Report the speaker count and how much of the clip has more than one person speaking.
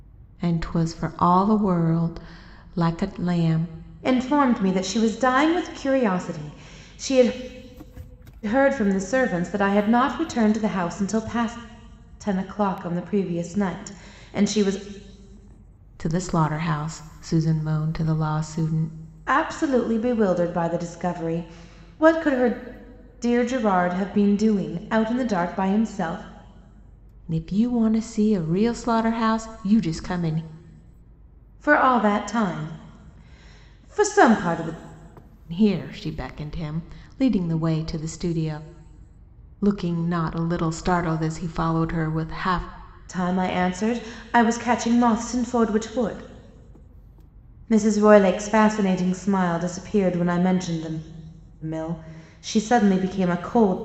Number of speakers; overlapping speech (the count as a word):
two, no overlap